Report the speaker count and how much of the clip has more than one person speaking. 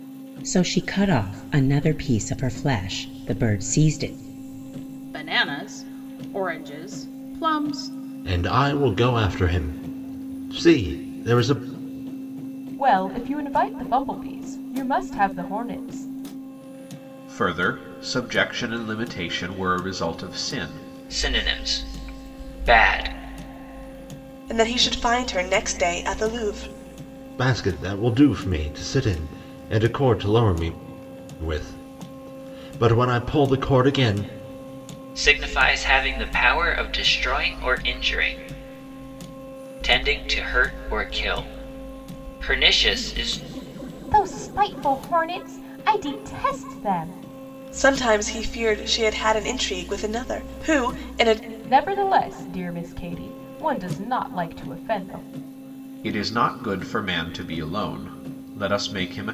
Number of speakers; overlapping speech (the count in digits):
7, no overlap